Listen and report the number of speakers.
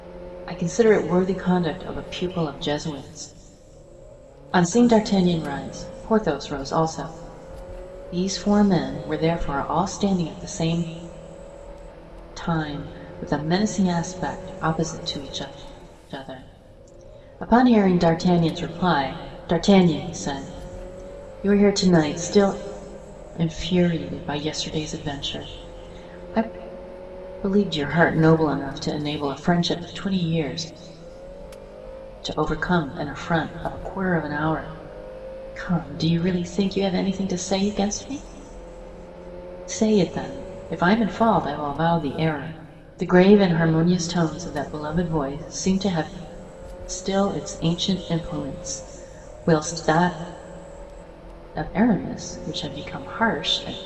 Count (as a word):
one